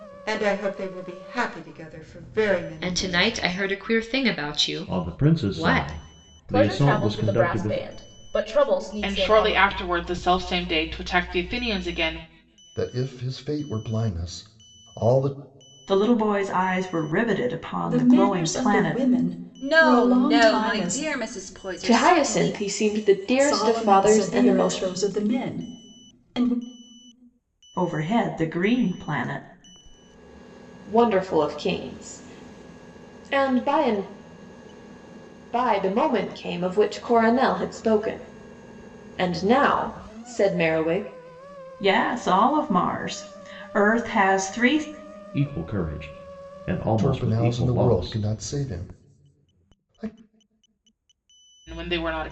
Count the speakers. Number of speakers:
10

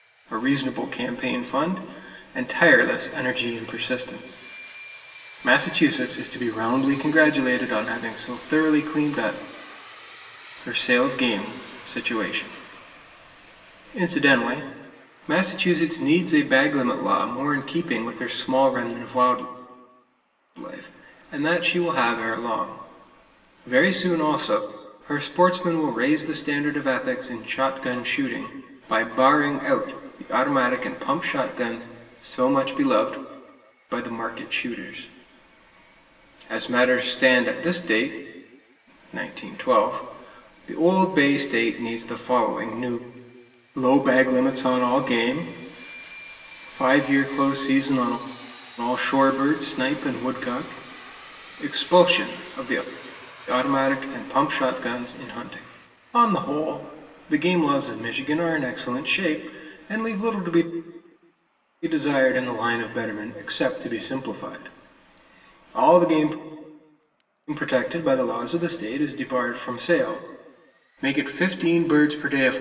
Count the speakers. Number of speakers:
1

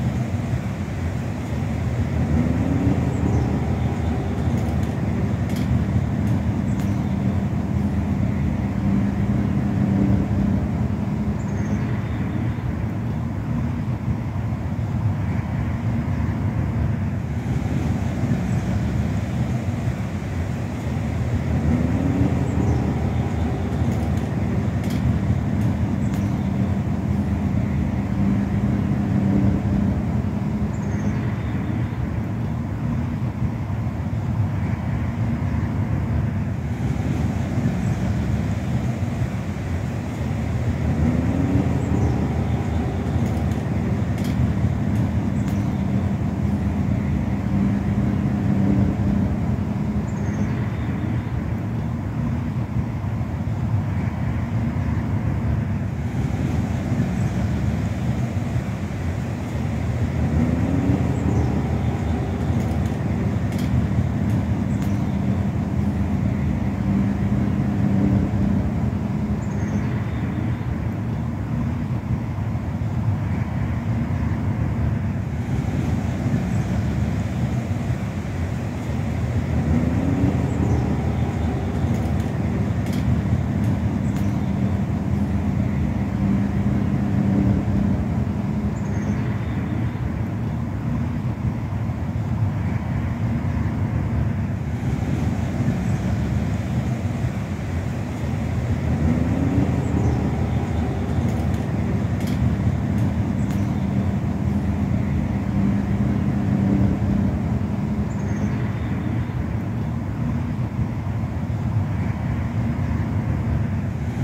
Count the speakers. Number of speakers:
0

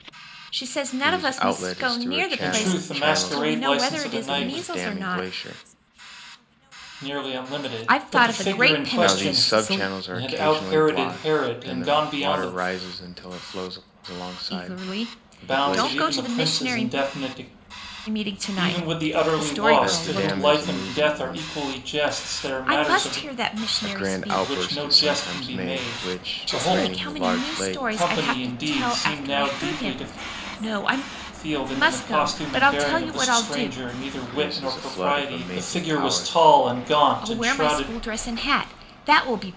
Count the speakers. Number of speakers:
3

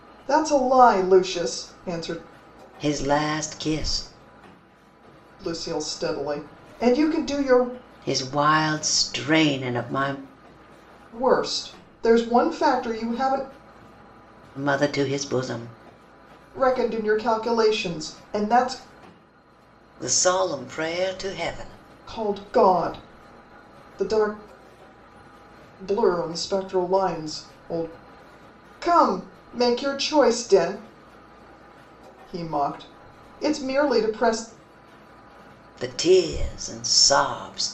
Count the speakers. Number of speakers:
2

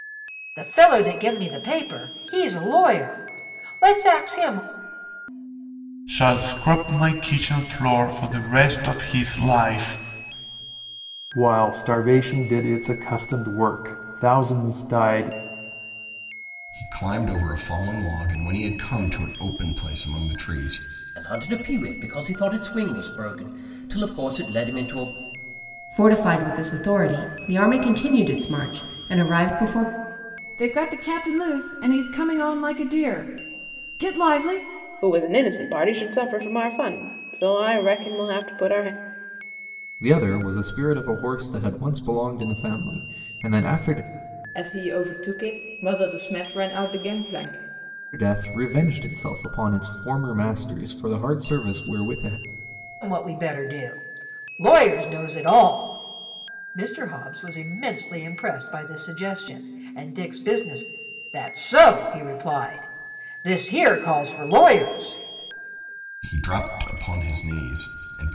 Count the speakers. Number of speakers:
10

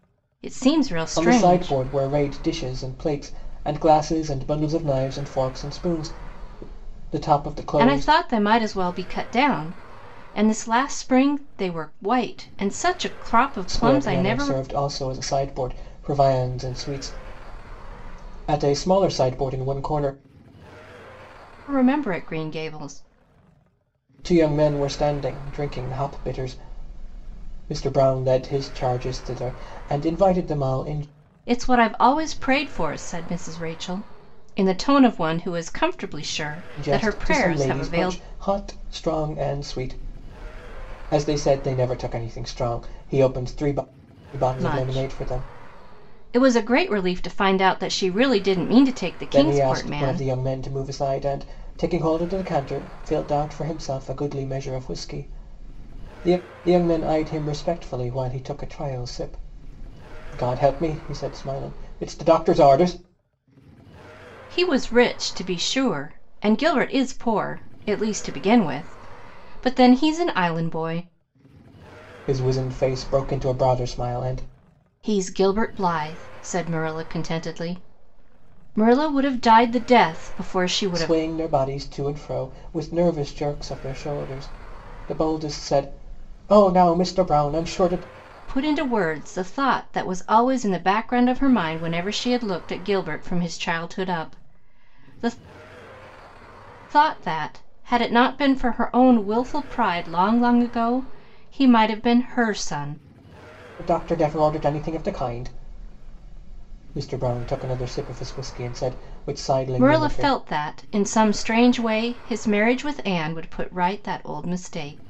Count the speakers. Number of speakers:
2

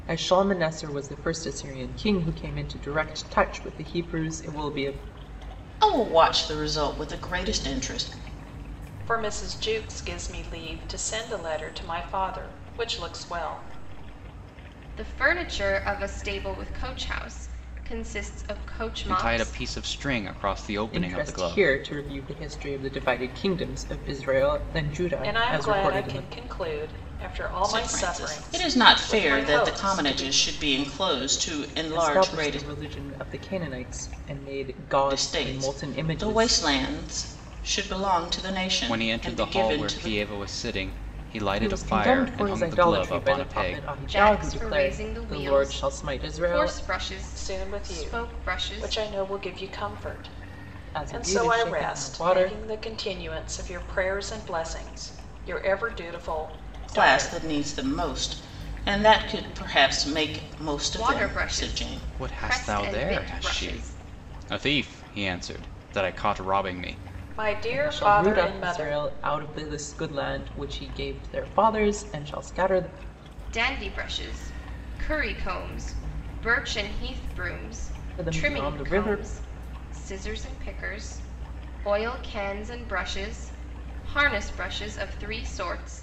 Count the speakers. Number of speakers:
5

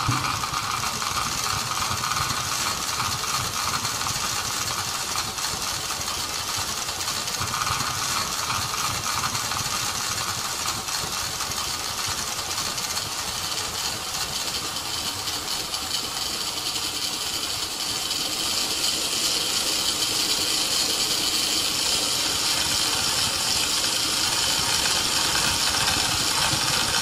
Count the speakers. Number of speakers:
0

